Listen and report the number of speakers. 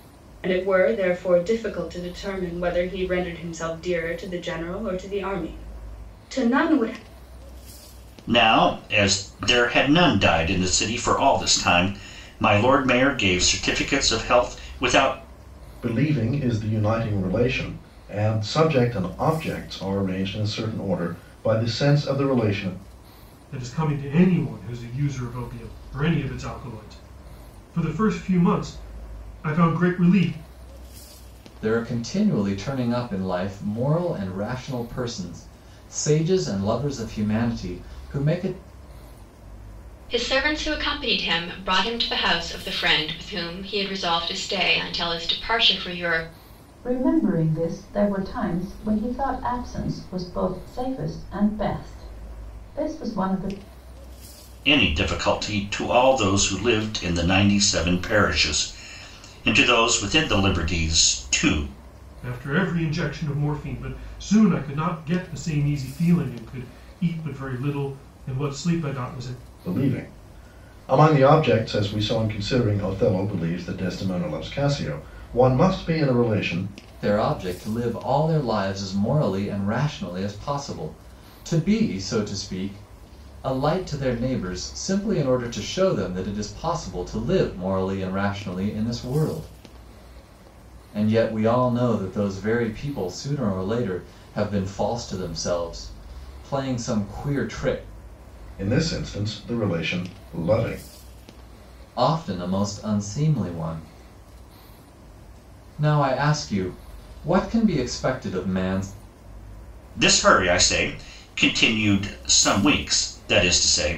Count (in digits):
7